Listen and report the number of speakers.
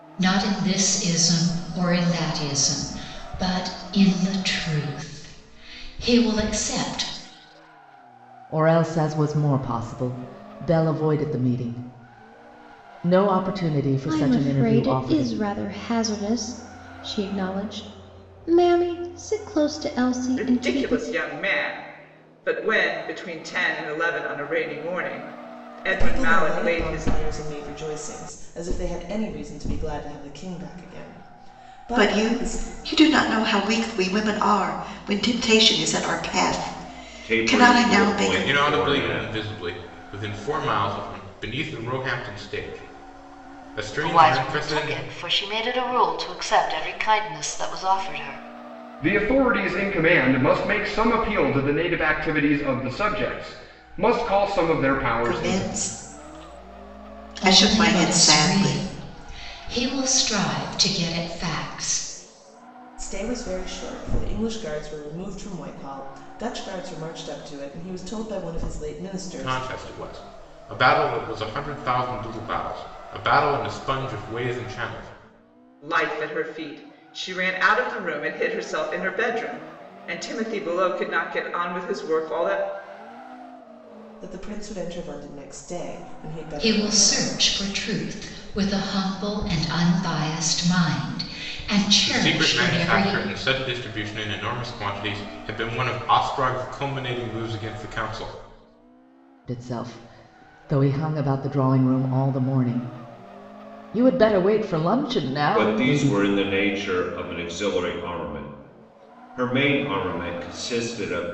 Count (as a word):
ten